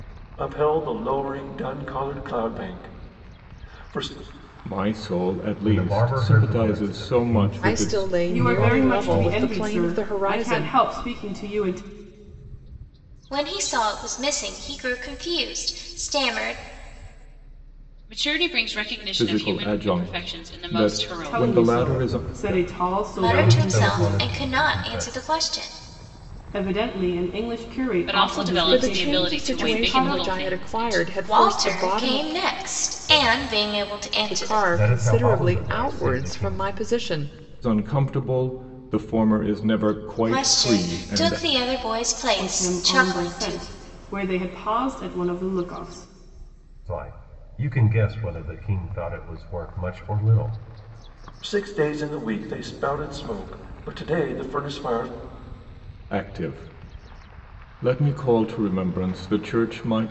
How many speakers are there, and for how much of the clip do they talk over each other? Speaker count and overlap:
7, about 36%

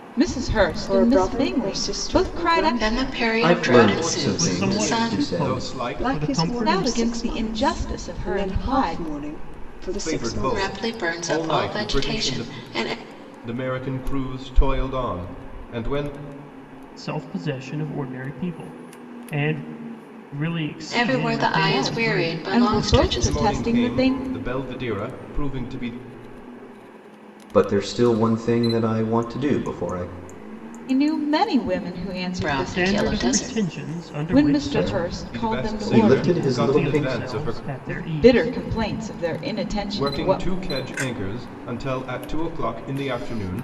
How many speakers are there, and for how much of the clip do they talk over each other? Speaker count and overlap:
6, about 46%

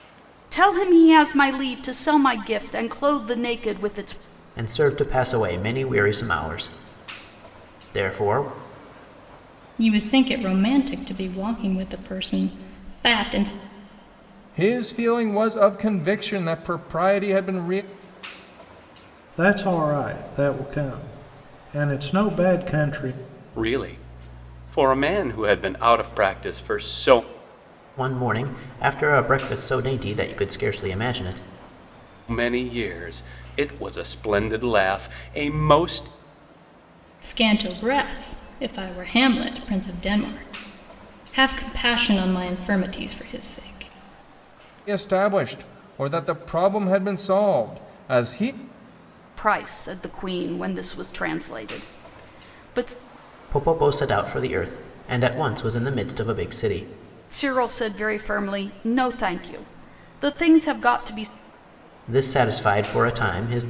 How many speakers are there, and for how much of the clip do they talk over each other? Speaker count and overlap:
6, no overlap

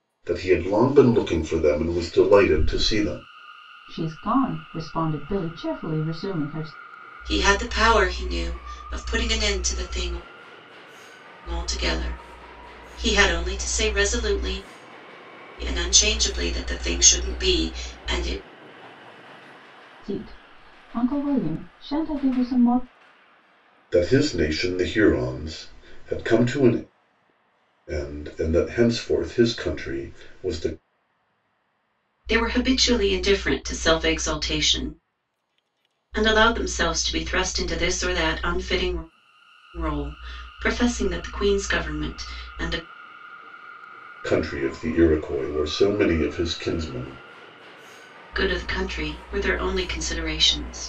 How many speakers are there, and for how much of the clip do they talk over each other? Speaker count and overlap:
3, no overlap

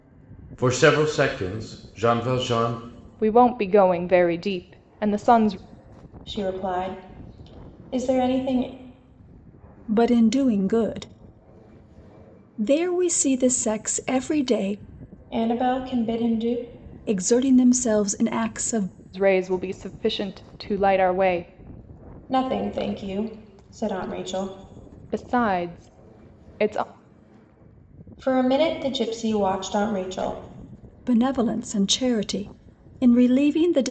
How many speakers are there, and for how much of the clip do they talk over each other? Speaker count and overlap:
4, no overlap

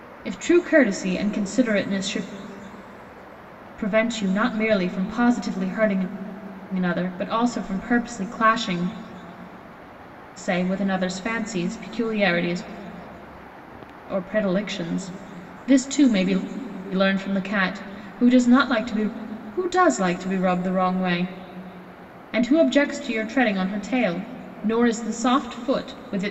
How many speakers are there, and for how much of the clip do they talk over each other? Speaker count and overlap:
1, no overlap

